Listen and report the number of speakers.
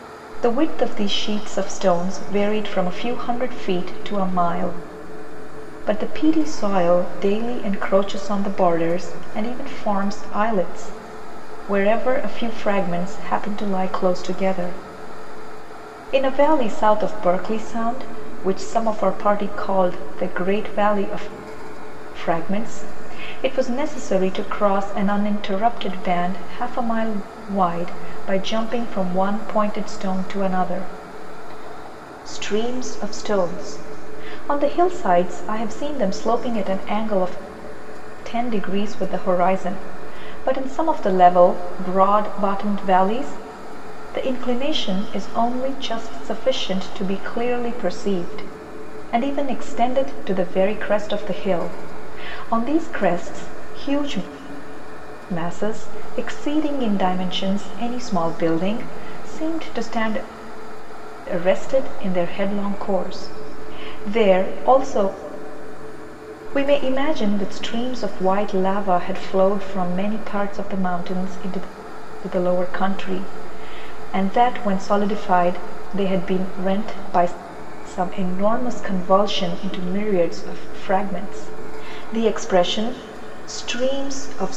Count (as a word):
one